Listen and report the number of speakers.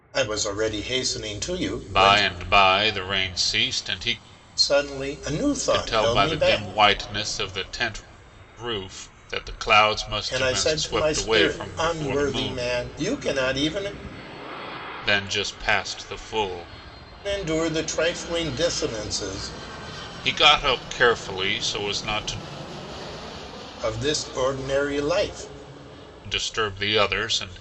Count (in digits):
2